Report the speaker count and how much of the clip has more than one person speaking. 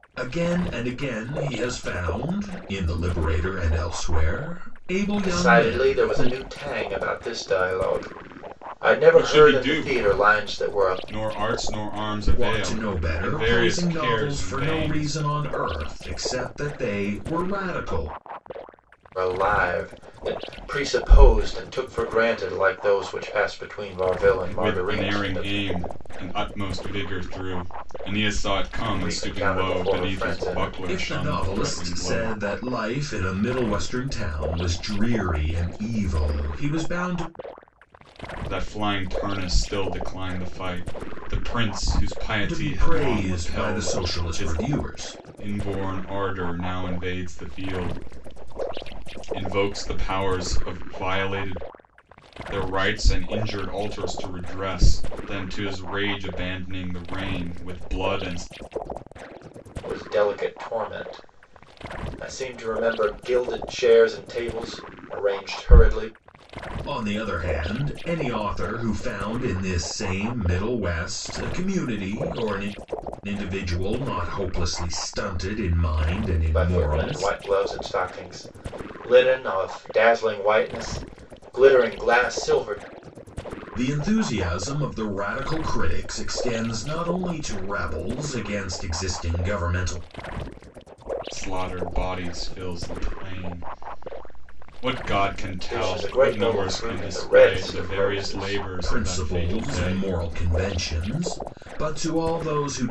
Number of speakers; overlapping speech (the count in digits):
3, about 17%